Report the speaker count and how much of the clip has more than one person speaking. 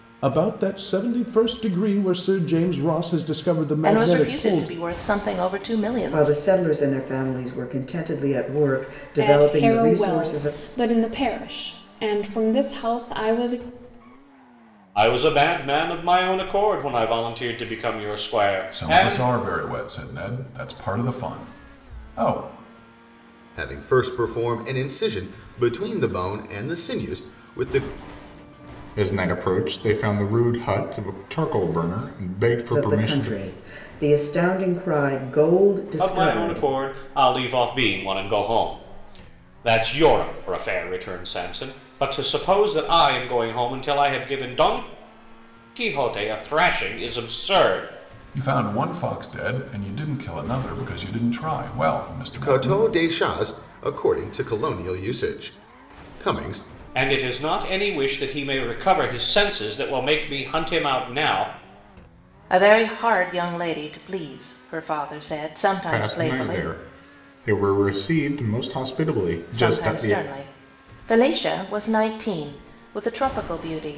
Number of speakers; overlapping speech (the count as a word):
eight, about 9%